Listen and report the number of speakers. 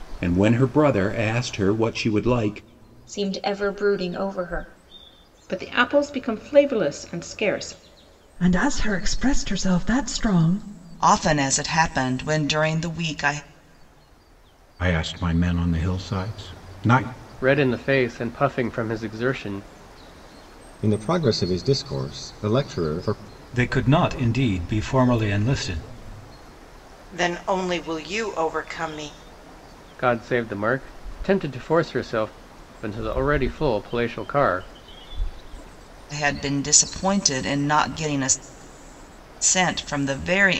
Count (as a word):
ten